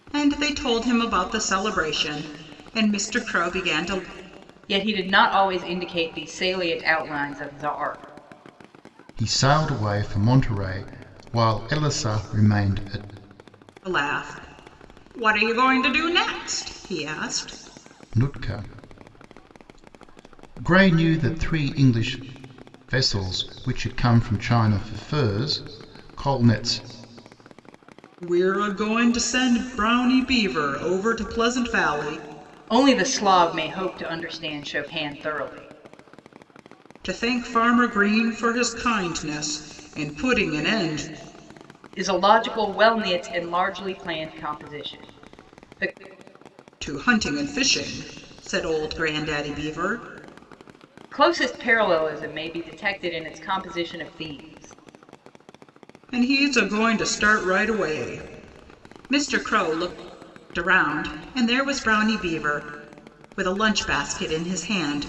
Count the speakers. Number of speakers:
three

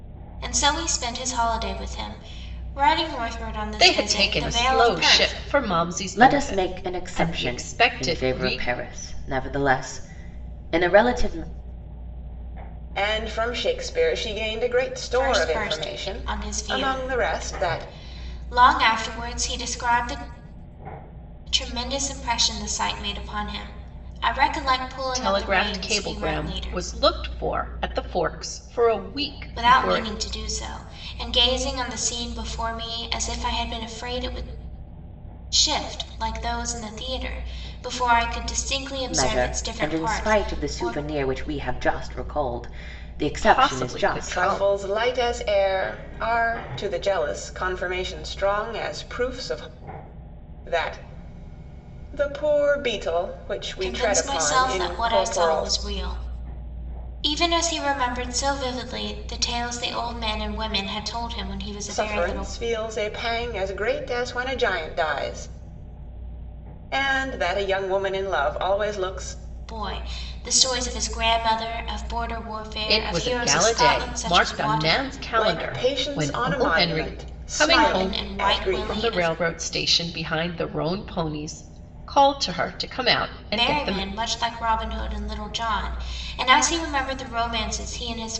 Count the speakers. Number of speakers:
four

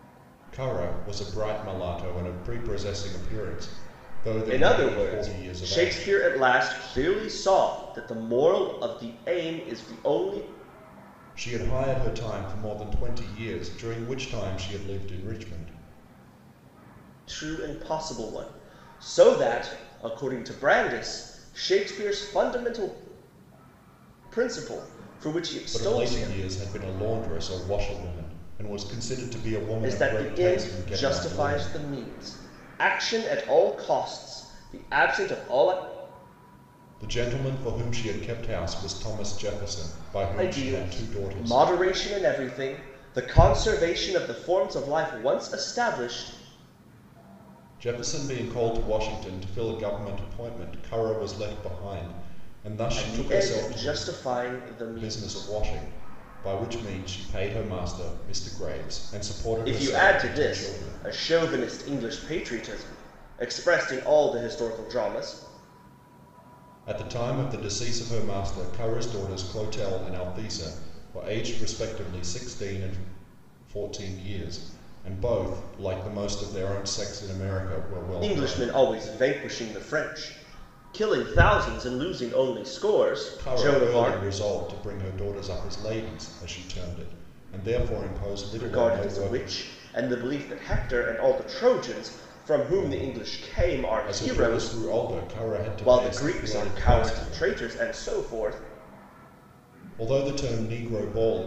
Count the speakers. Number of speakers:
two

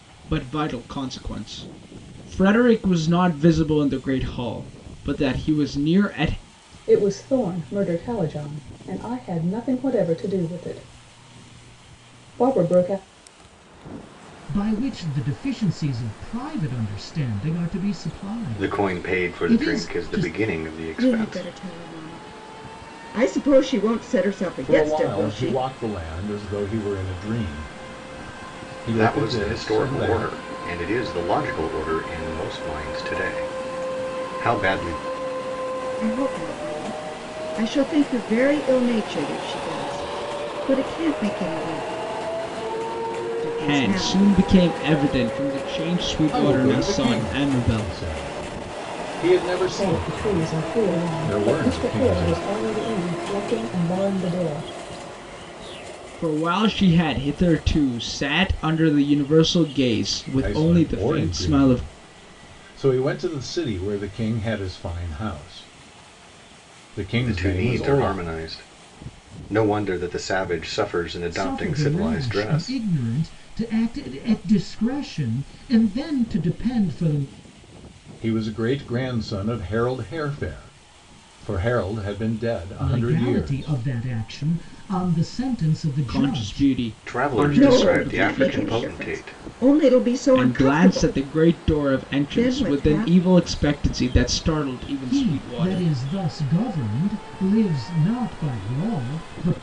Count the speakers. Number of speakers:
six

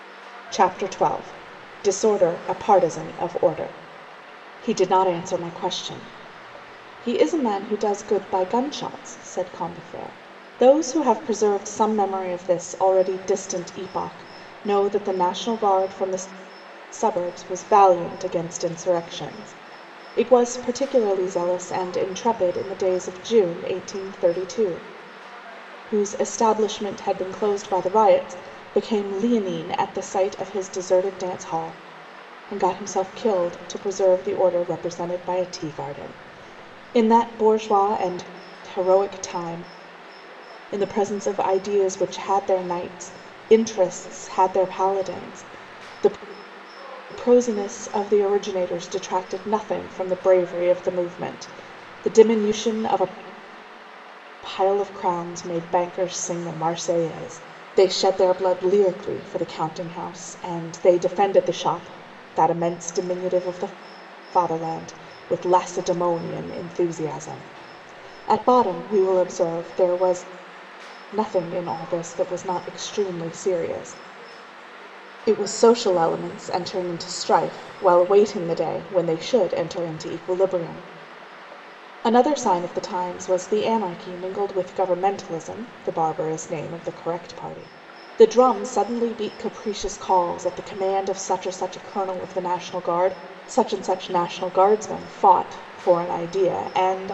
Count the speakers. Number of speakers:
one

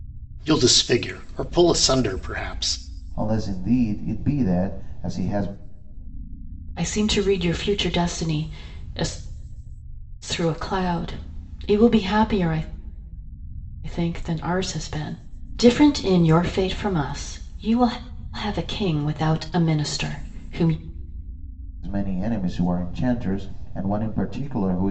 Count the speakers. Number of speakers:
three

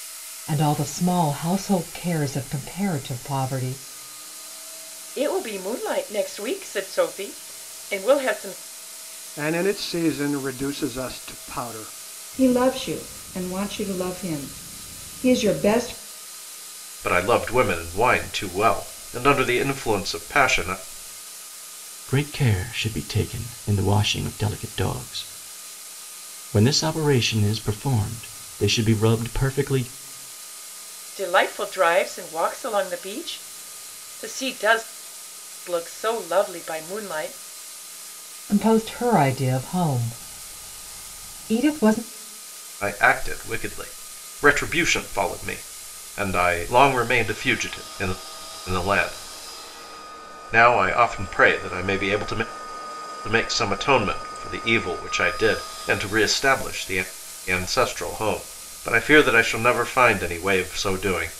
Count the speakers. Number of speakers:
six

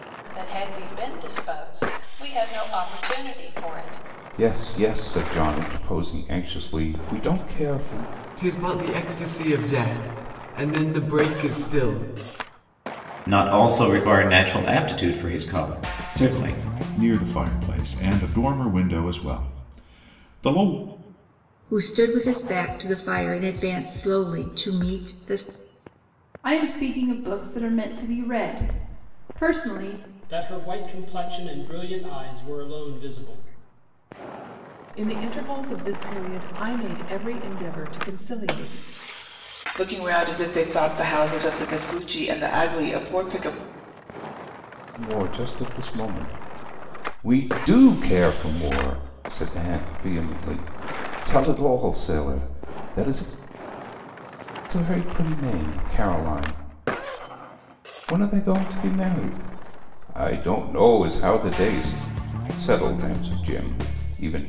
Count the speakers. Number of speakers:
ten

